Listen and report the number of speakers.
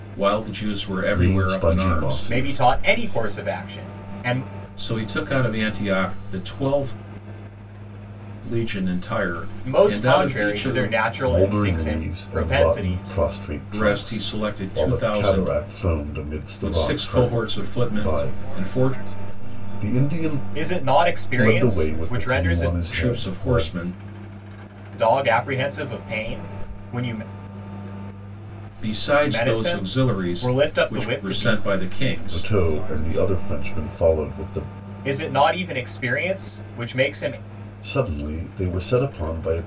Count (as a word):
four